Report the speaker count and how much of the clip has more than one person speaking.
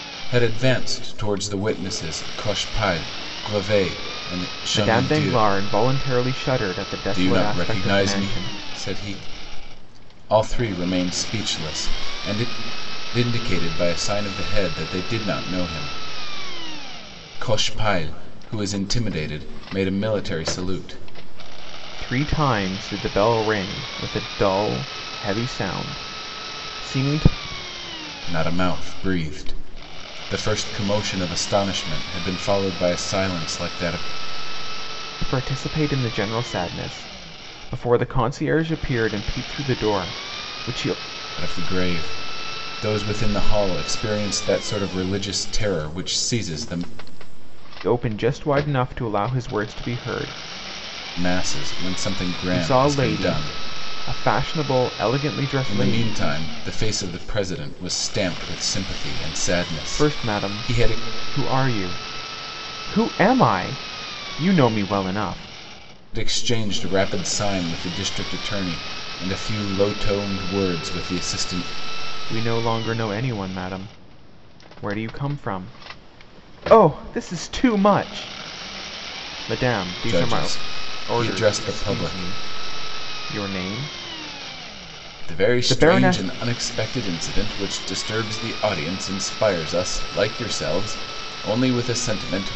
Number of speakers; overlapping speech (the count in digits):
2, about 8%